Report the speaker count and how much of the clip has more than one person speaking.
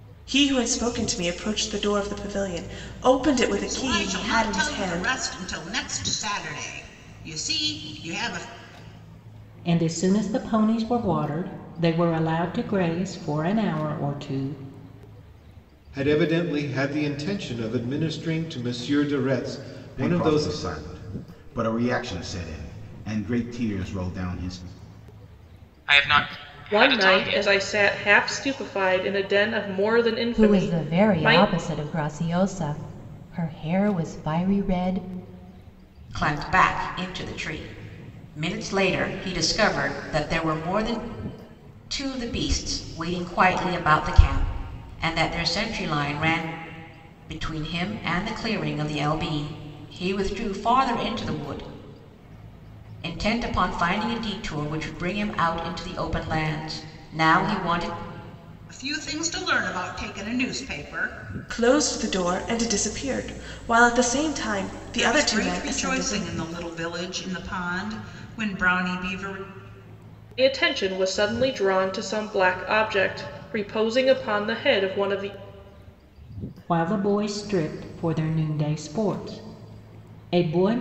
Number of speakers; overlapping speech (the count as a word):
nine, about 7%